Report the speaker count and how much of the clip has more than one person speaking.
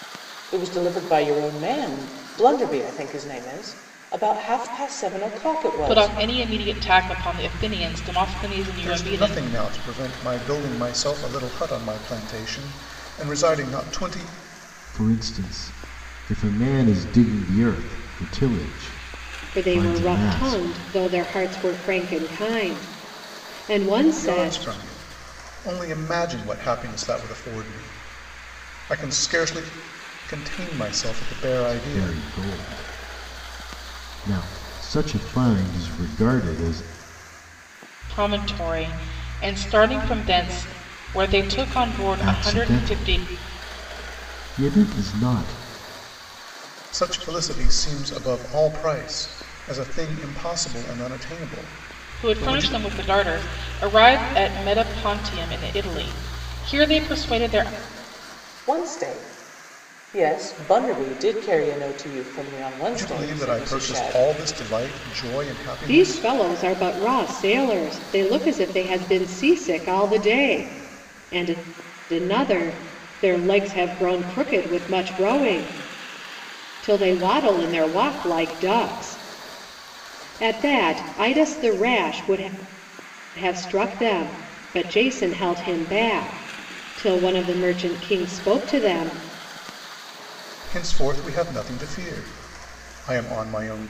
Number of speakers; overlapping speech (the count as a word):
five, about 7%